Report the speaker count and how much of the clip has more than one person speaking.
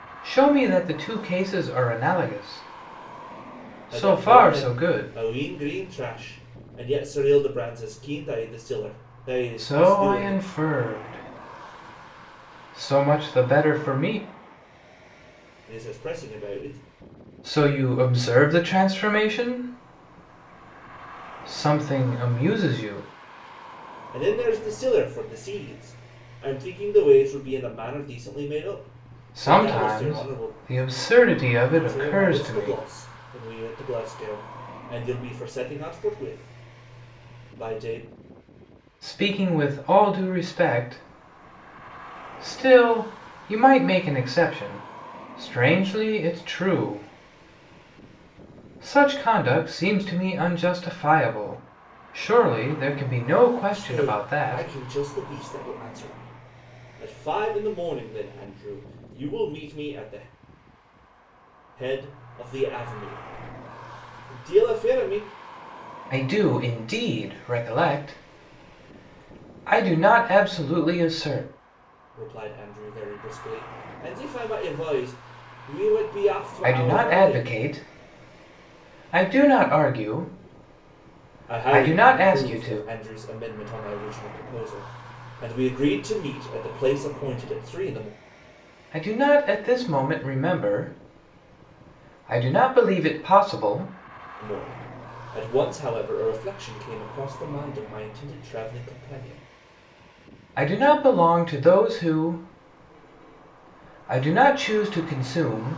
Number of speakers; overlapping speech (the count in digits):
2, about 7%